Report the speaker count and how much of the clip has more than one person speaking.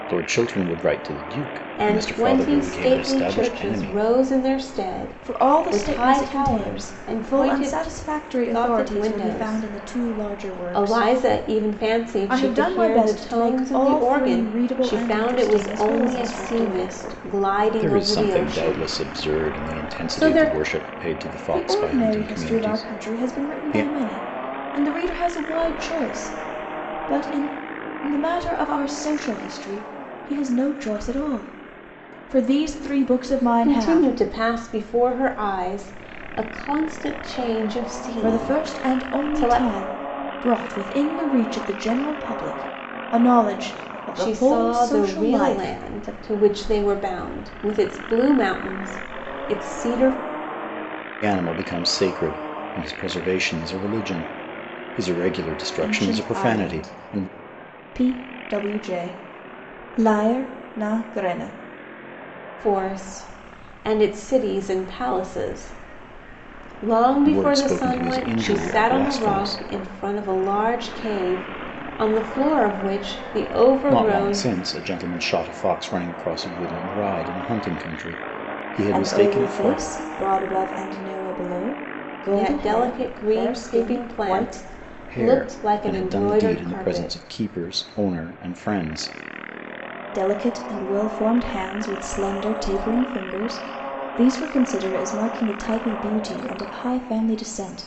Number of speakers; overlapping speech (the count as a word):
three, about 32%